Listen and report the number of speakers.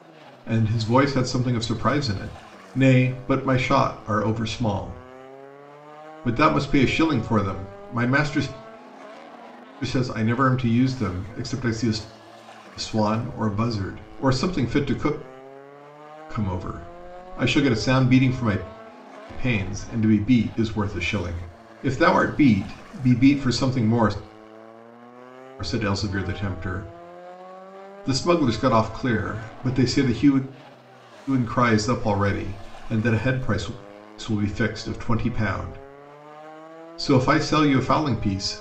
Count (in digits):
1